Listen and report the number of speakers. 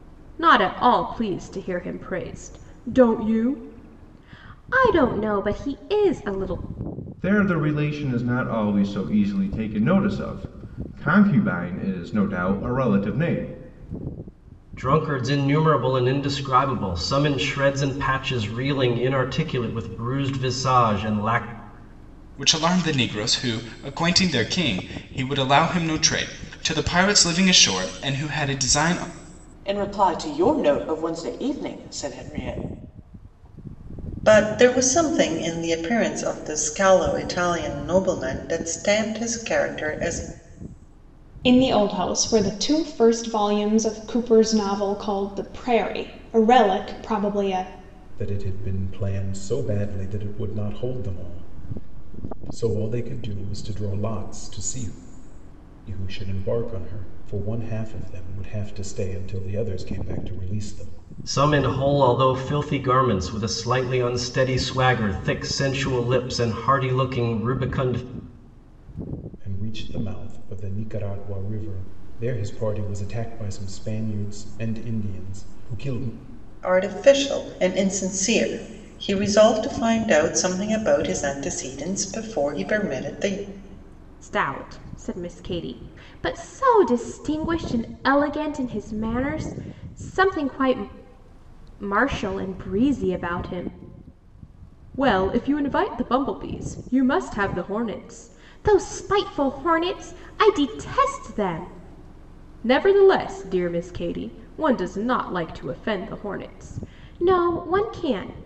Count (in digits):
8